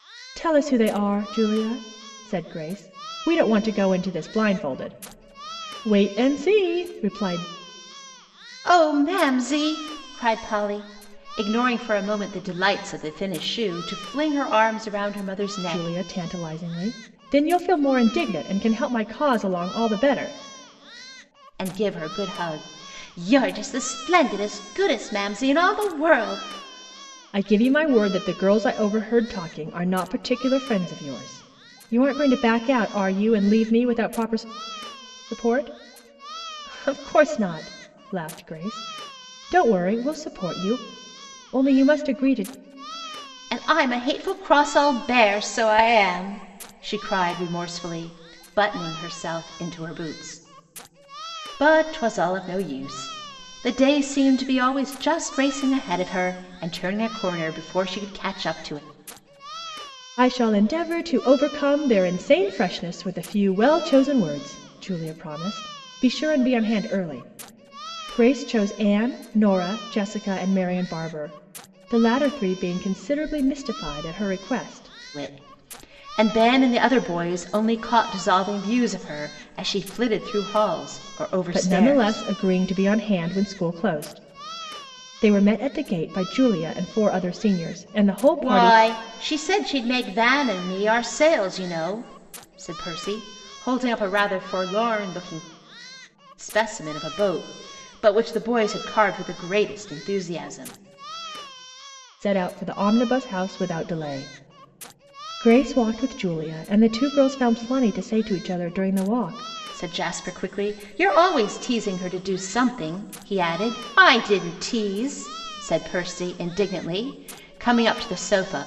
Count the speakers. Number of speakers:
two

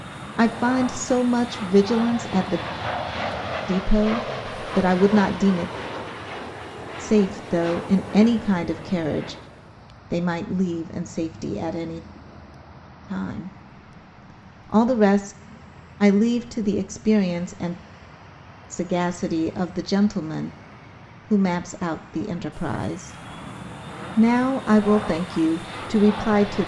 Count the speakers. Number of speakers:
one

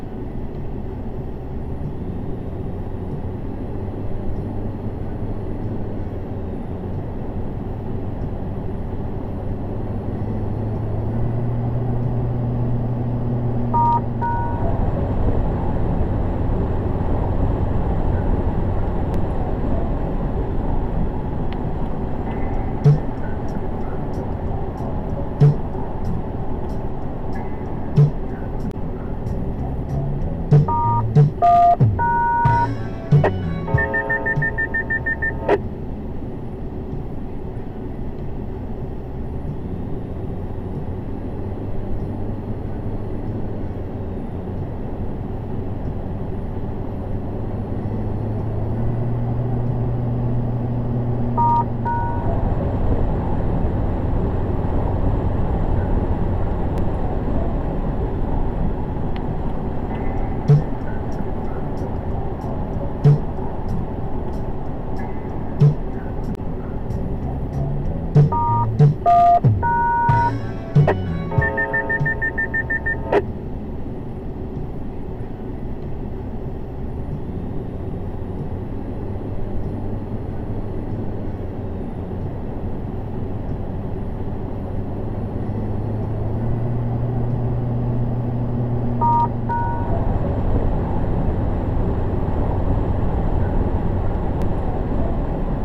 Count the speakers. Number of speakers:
zero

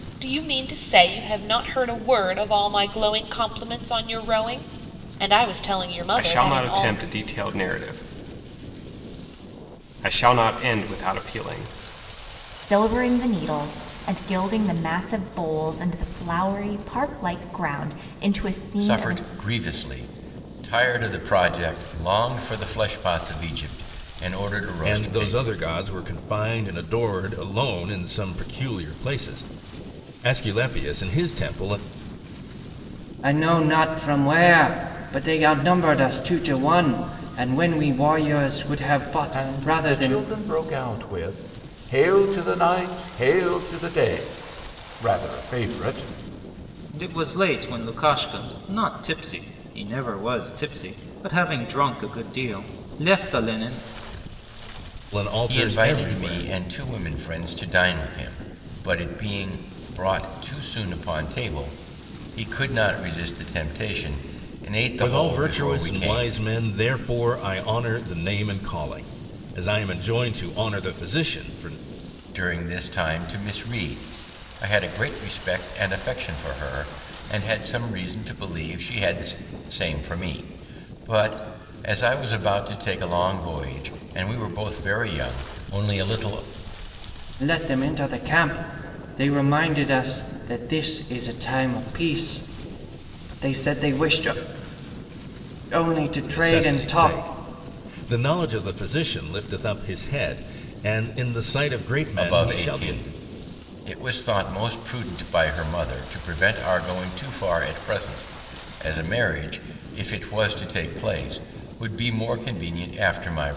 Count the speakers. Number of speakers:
eight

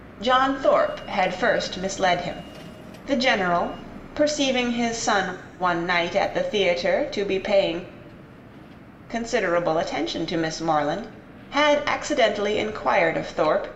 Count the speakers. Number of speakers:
one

